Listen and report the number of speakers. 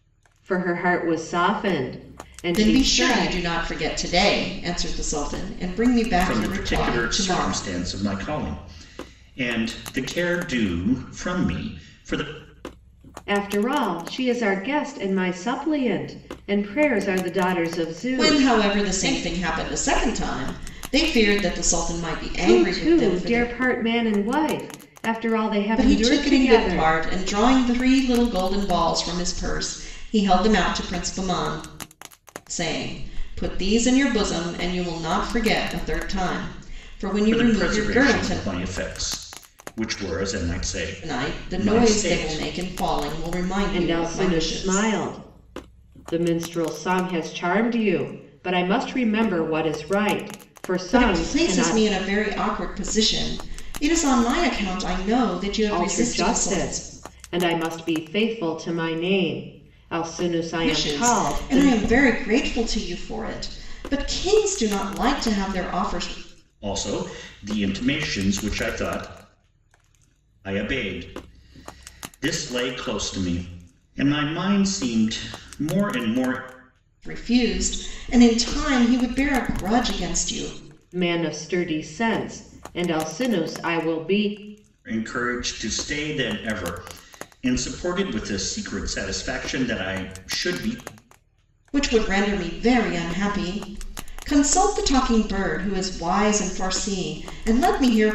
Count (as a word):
three